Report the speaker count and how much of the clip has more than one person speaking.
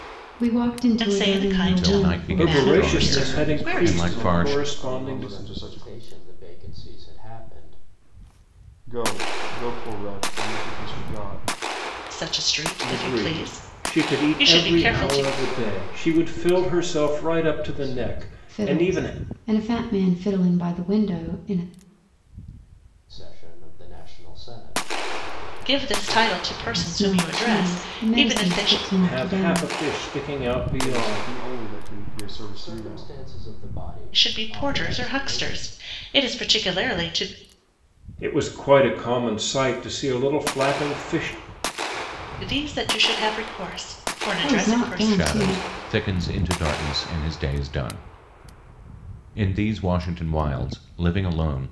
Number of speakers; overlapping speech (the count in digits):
6, about 36%